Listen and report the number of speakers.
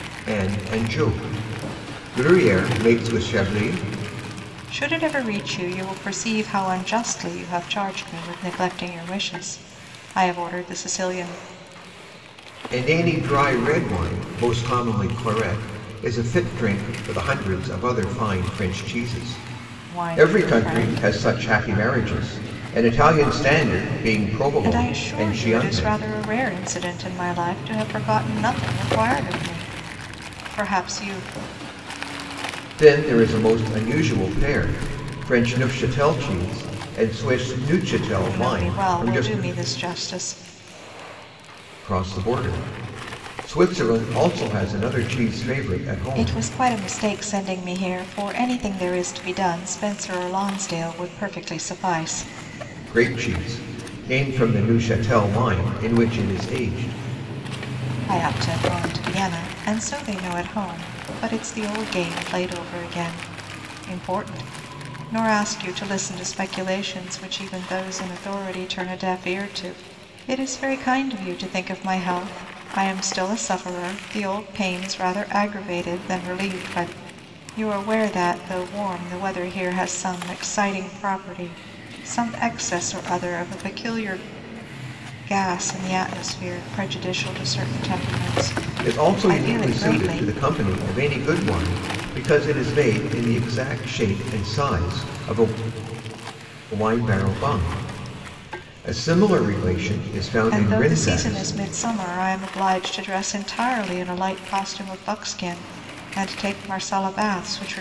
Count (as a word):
two